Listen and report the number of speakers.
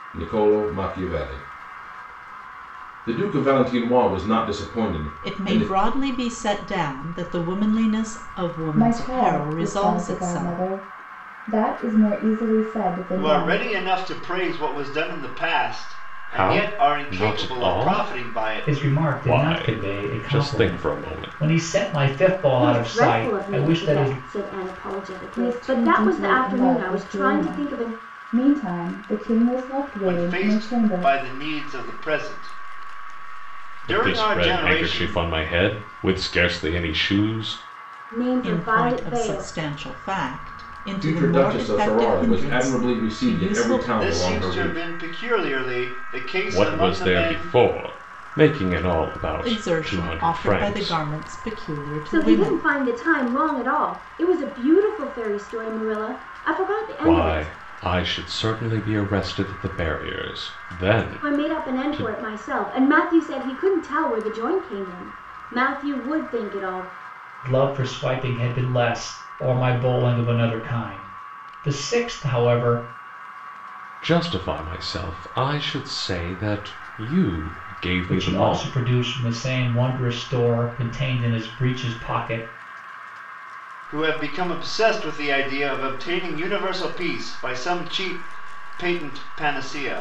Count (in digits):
7